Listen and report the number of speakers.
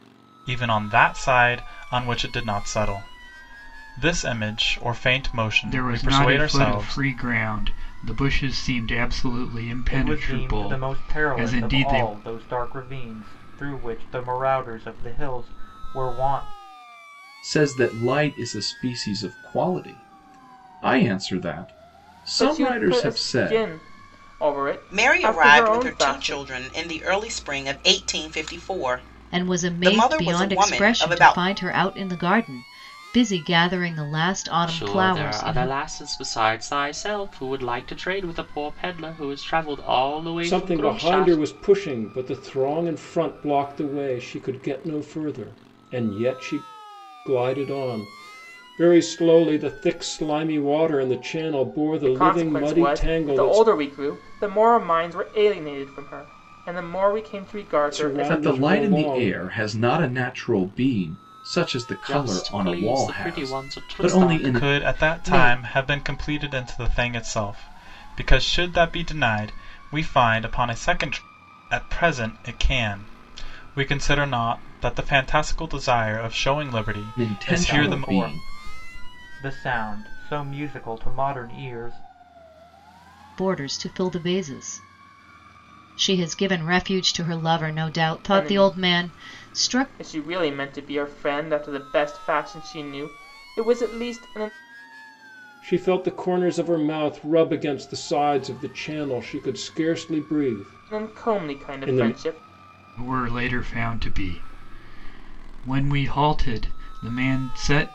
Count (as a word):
nine